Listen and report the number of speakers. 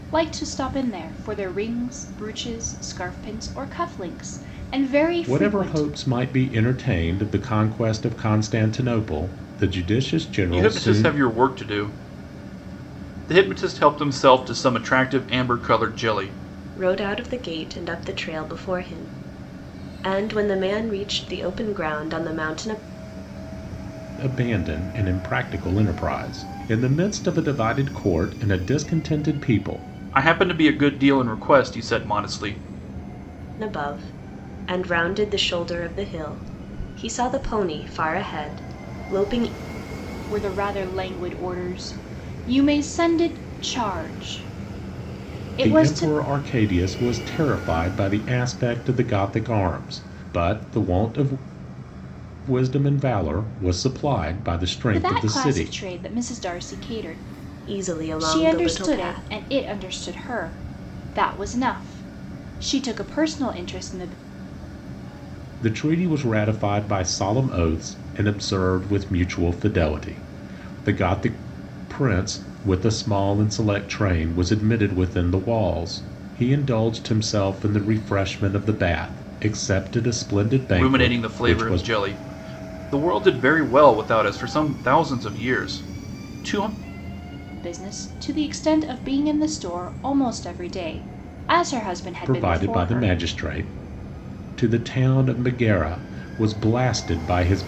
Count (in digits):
4